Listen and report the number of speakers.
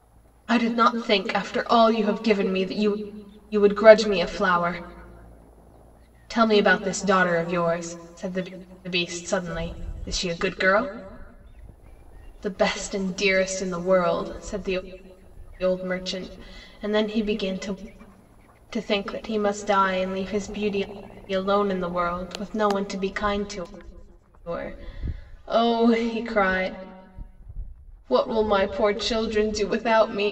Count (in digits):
1